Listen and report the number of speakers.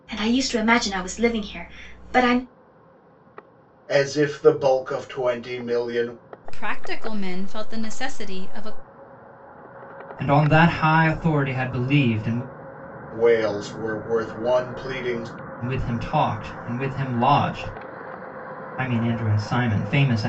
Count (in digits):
4